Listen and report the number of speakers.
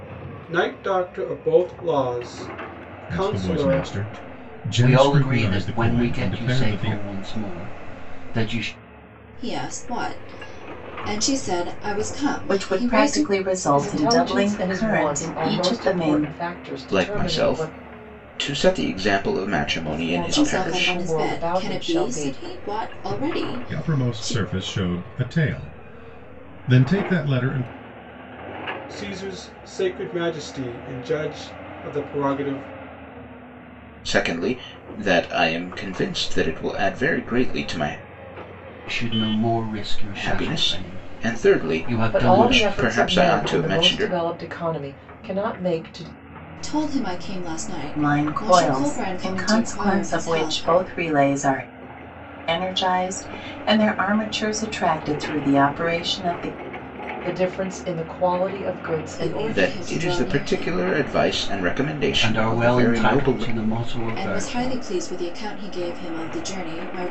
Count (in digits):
7